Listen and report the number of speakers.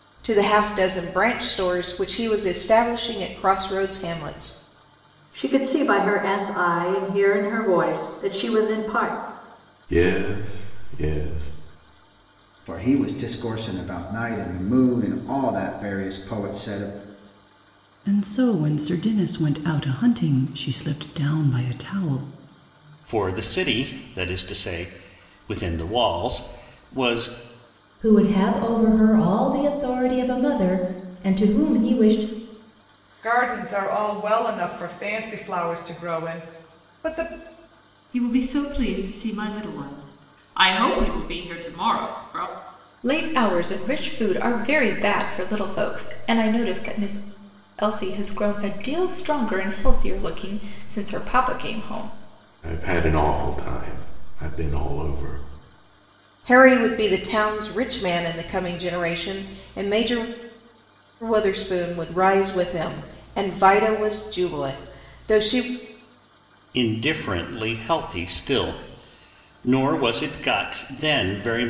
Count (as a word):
ten